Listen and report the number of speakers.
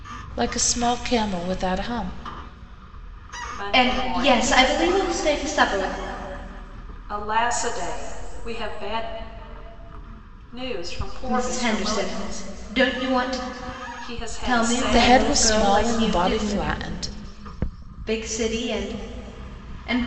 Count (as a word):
three